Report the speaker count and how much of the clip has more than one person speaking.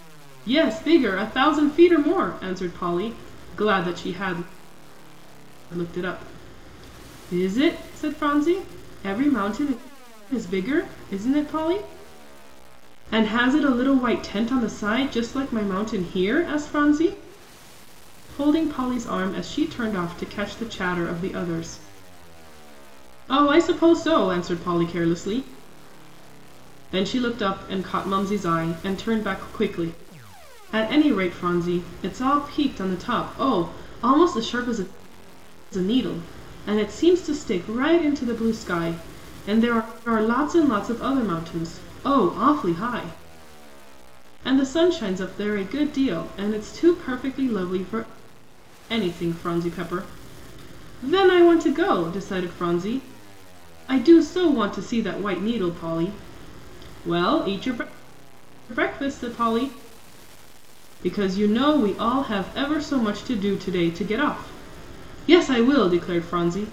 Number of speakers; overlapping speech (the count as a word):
one, no overlap